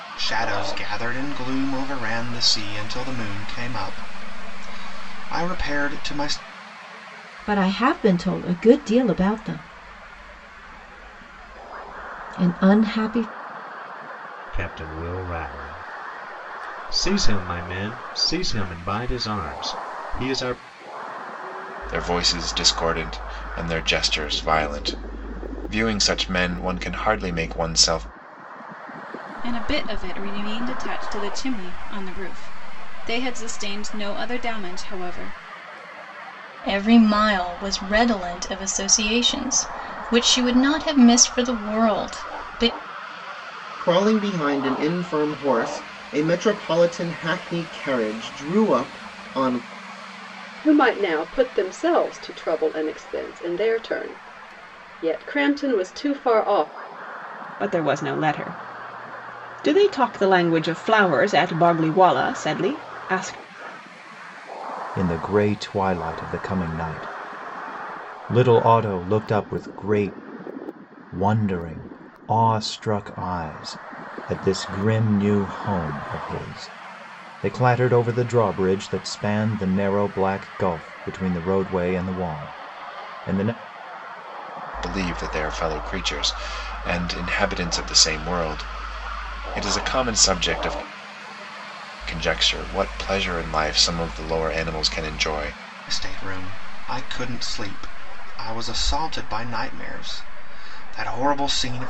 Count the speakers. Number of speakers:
10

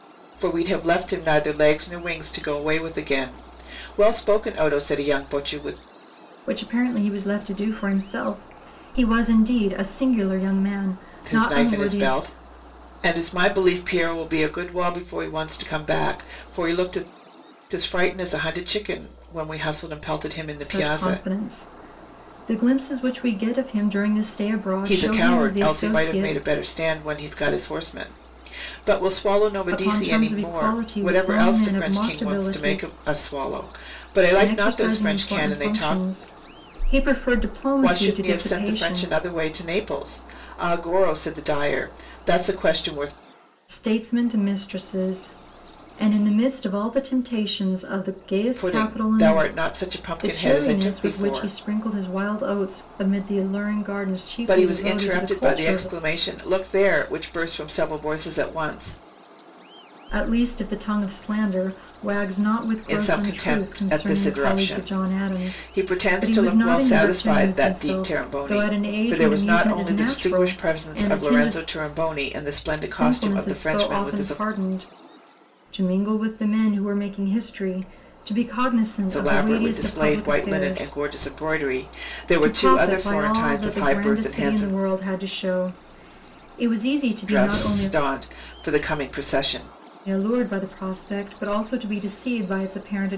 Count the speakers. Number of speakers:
2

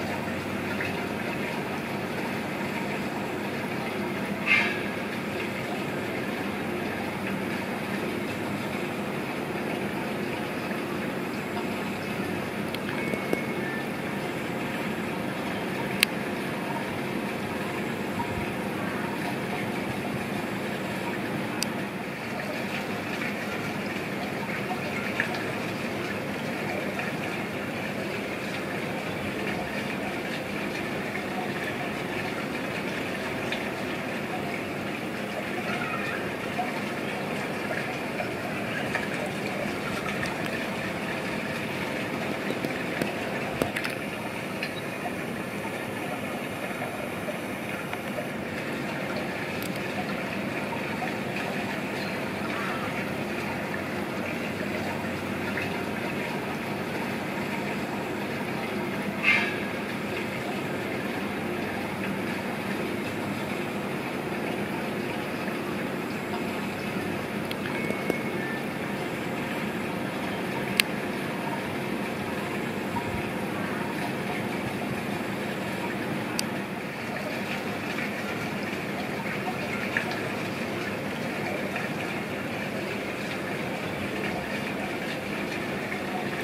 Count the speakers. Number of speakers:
0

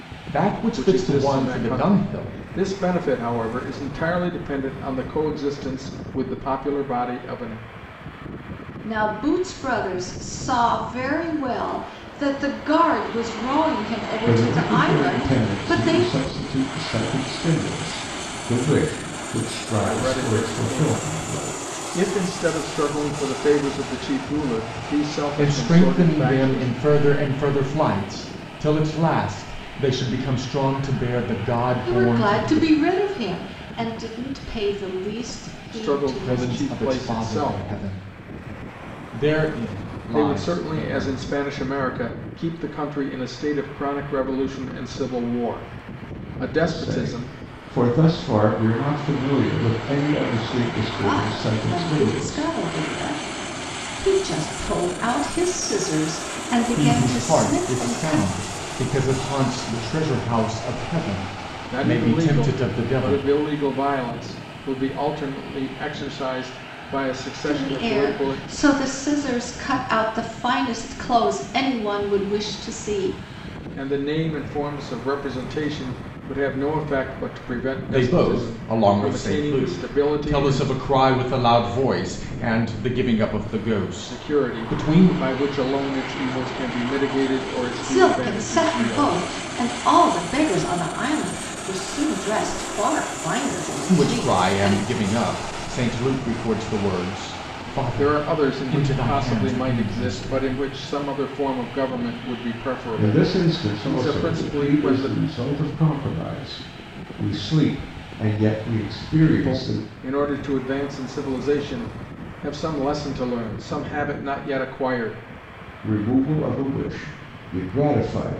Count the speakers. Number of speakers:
4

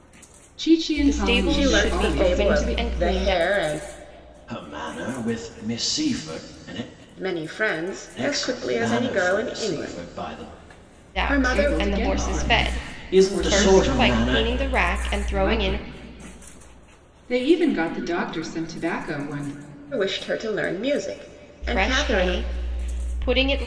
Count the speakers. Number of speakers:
4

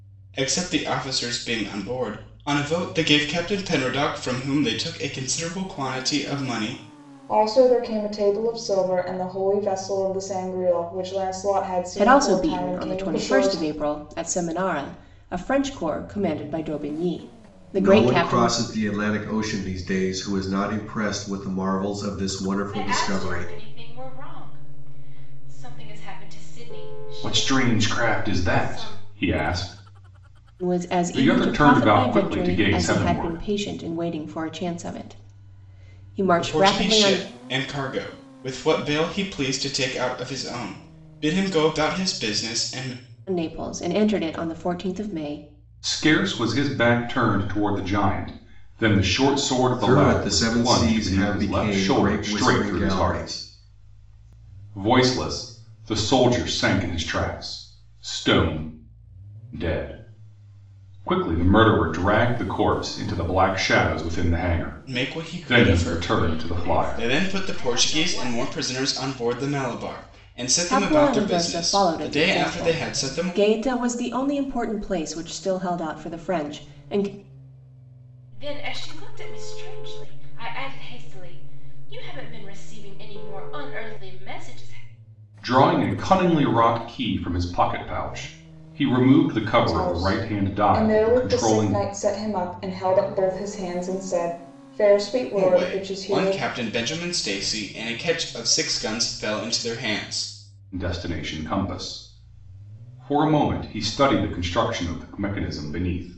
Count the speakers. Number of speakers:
6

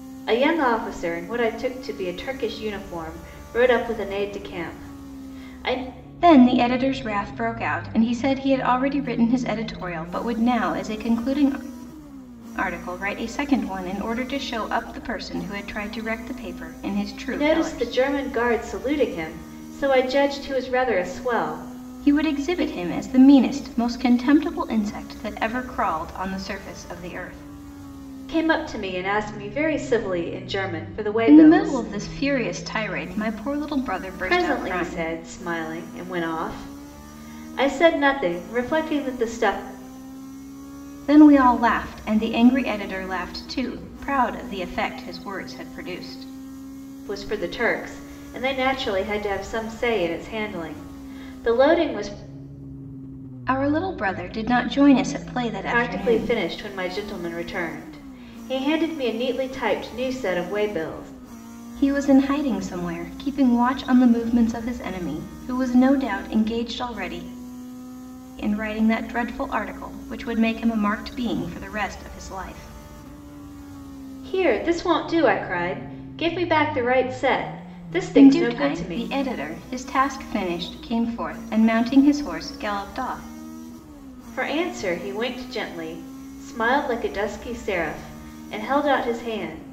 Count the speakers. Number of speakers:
2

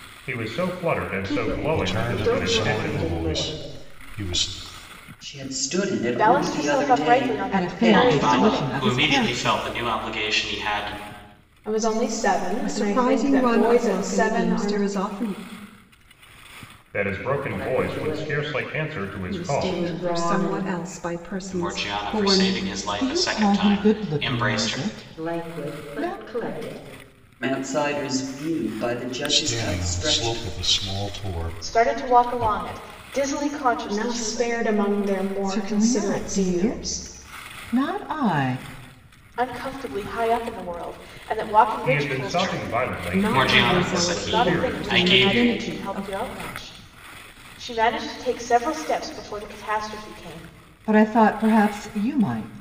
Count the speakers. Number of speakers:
9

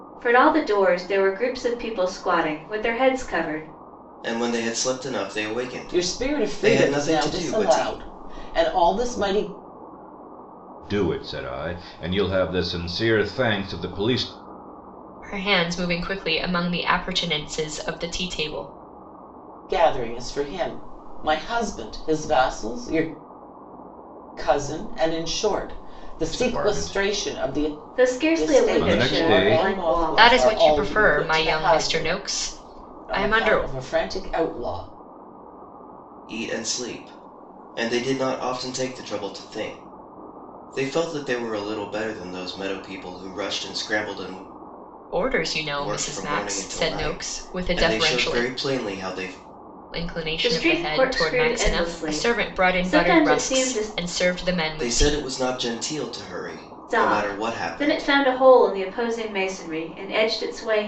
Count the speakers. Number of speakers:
5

